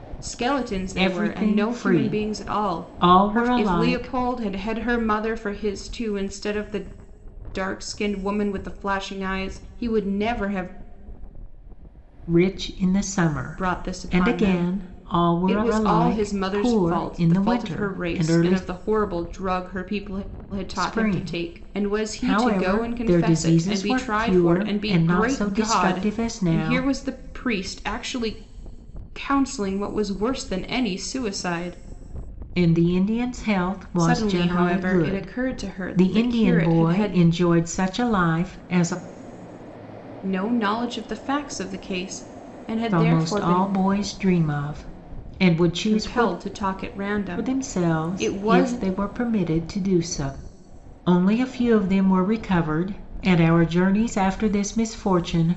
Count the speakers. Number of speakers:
two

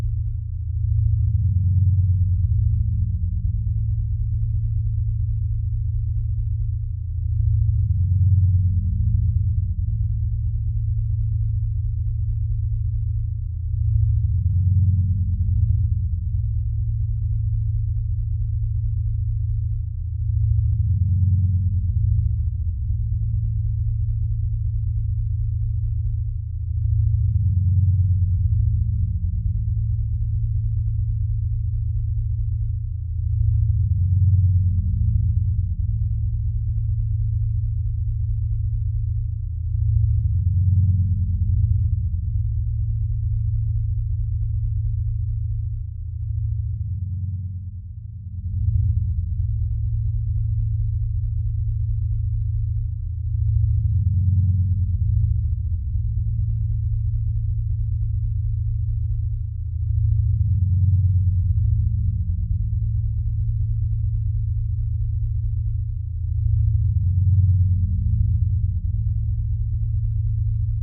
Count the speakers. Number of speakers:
zero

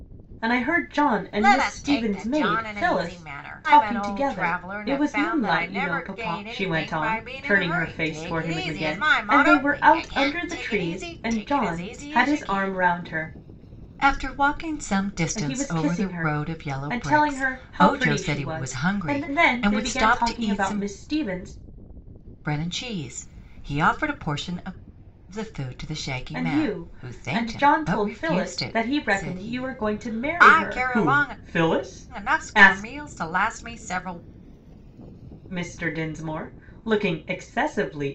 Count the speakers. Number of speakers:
two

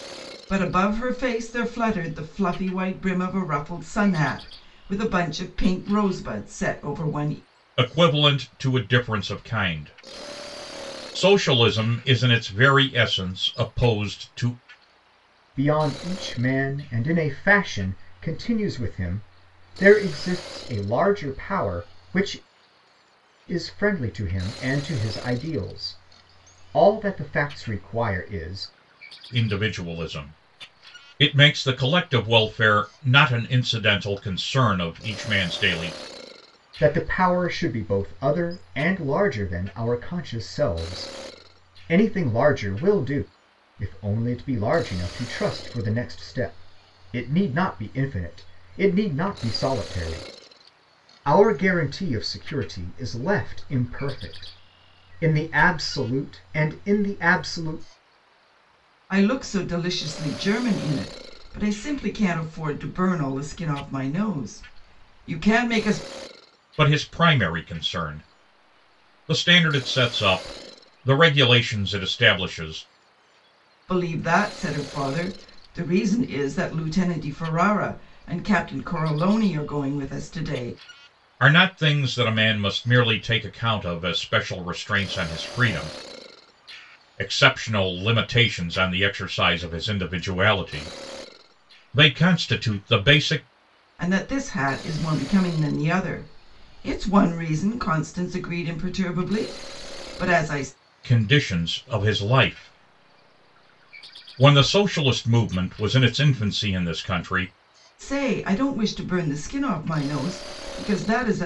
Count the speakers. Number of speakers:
three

